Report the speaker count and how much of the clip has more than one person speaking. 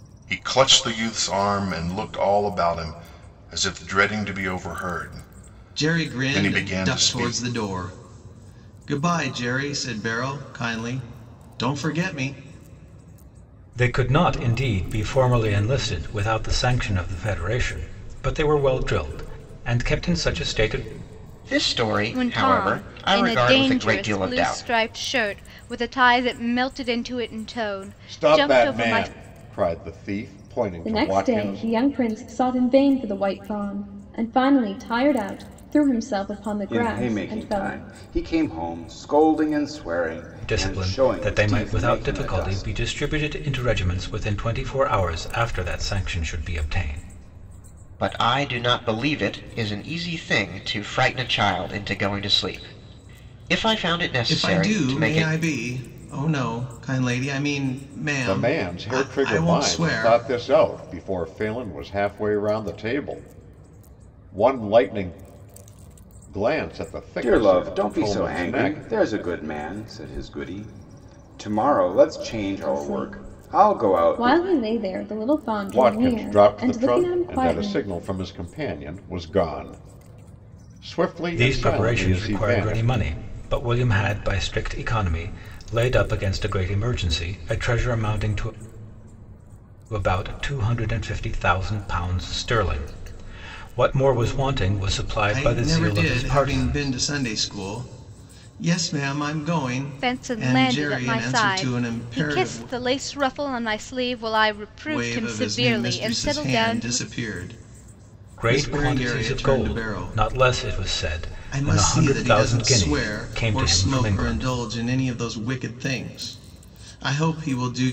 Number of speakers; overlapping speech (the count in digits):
8, about 27%